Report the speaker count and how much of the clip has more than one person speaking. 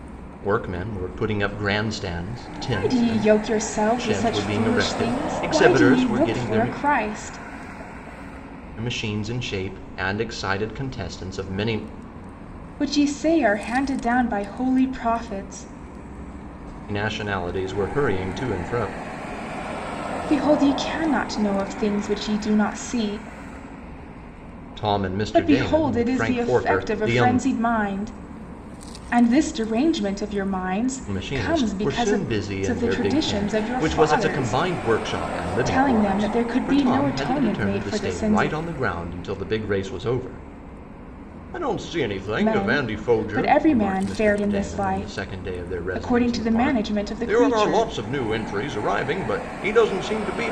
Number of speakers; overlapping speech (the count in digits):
2, about 33%